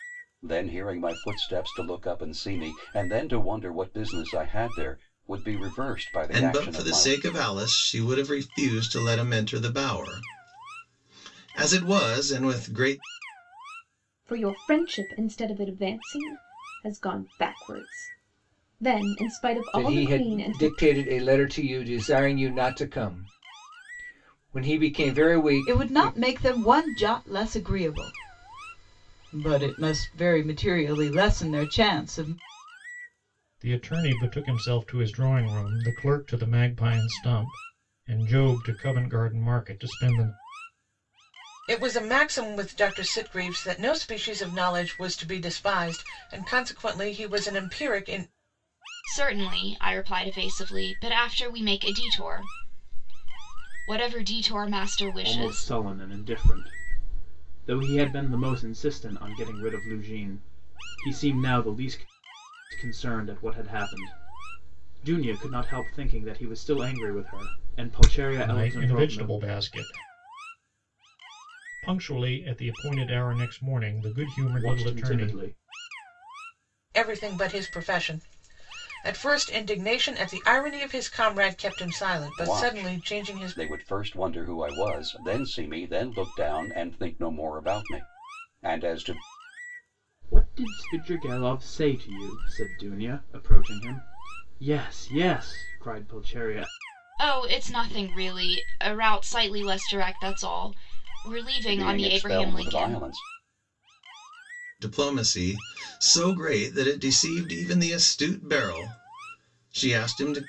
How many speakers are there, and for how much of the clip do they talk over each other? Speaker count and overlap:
9, about 7%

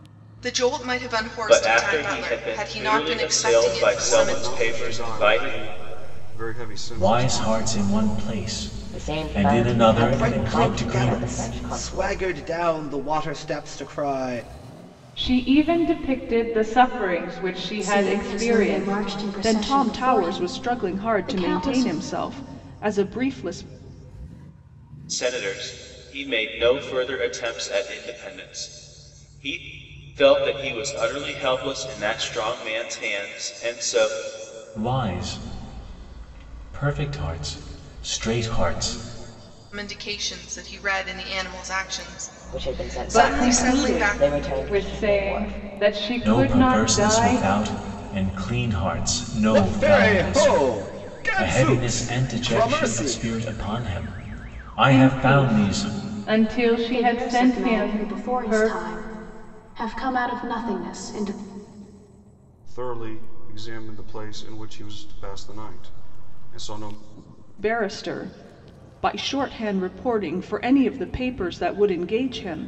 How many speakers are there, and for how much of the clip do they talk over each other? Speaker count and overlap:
9, about 32%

